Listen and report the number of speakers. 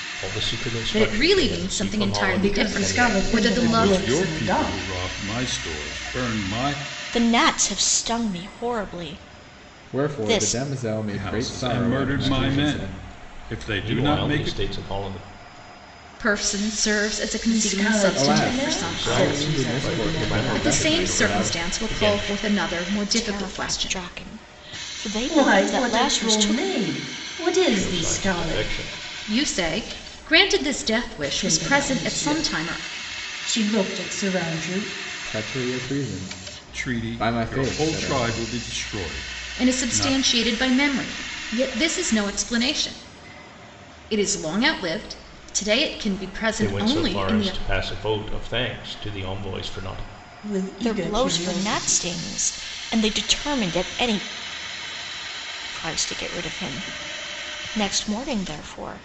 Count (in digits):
6